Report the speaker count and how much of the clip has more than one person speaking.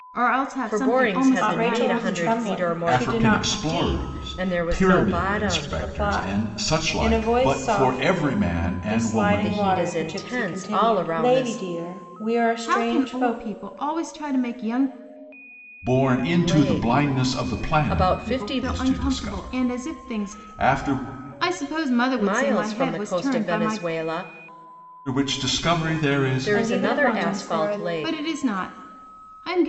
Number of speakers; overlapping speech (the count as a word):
four, about 66%